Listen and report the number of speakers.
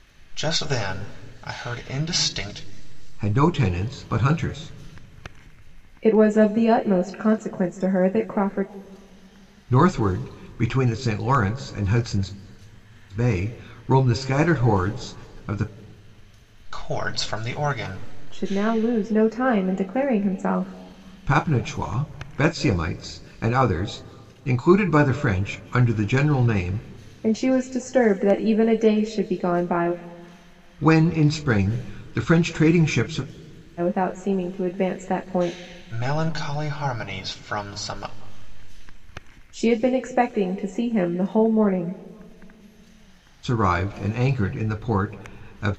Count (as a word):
three